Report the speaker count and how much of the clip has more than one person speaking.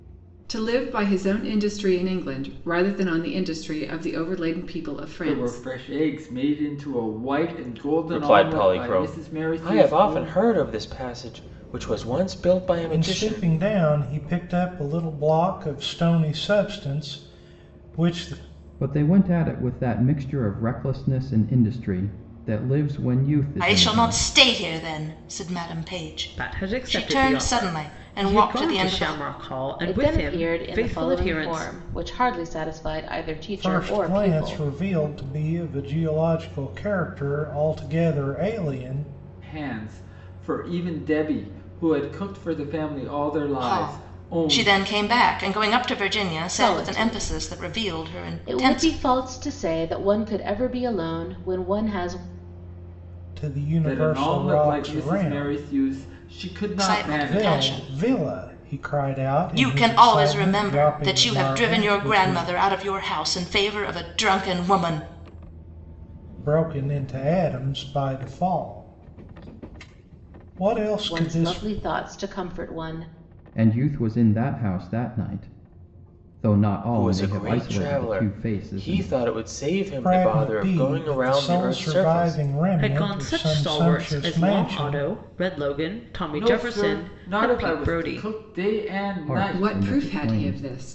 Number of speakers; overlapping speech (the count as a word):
eight, about 34%